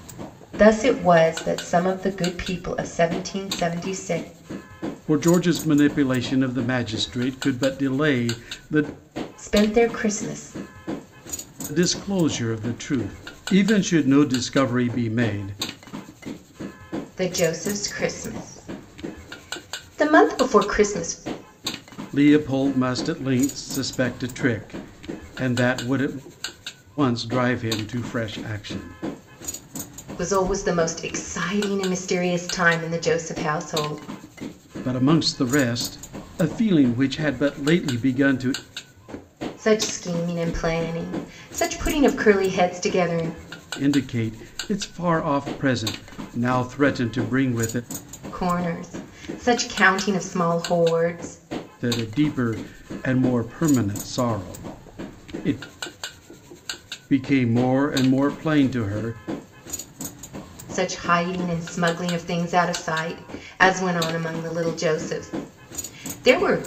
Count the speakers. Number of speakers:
two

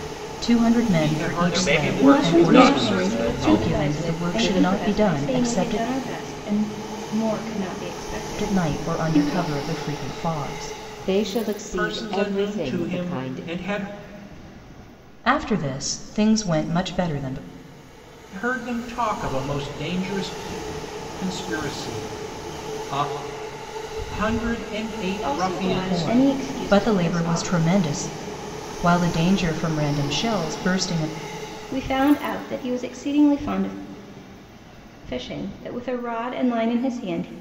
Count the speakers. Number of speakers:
five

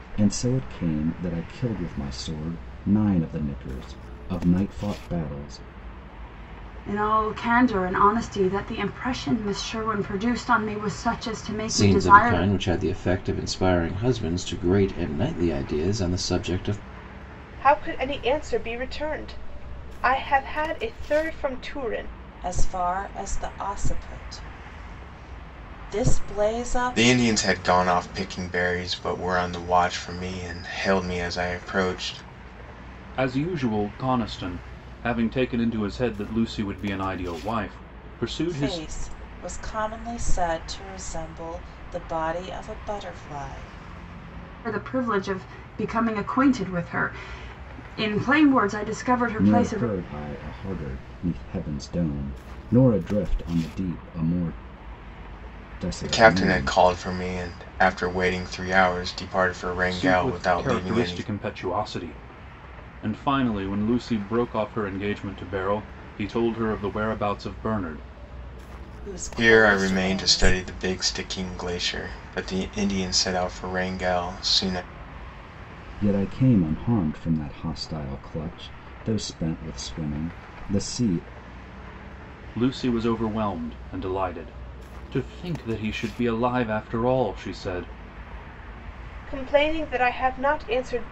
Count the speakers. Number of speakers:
seven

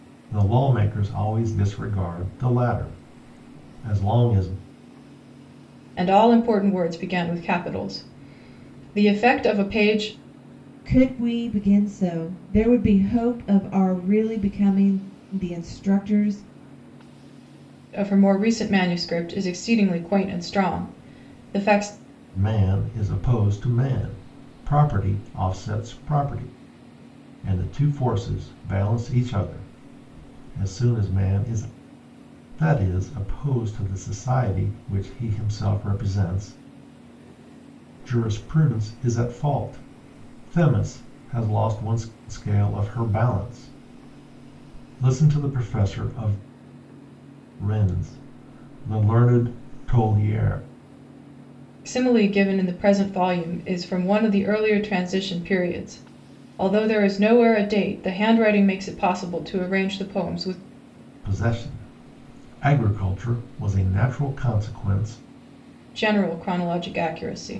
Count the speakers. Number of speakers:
three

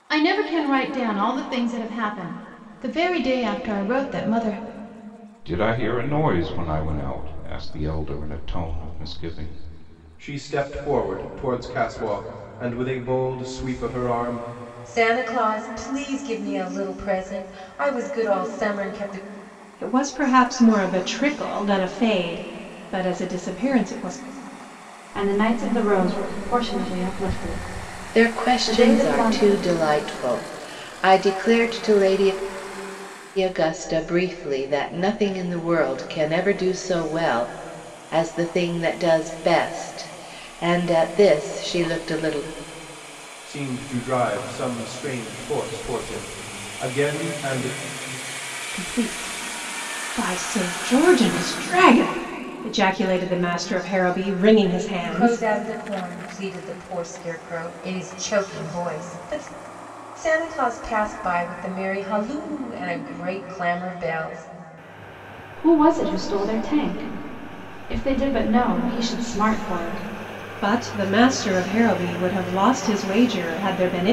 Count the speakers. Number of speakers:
seven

